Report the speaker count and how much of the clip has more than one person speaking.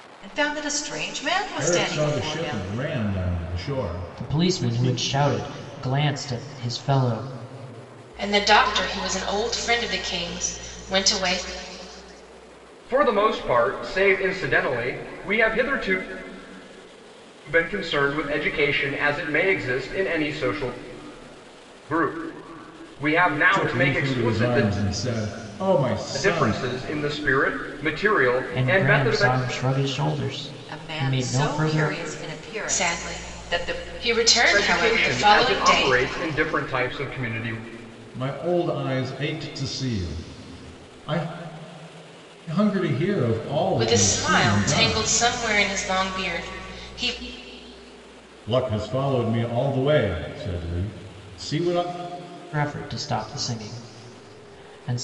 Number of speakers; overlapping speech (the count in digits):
5, about 18%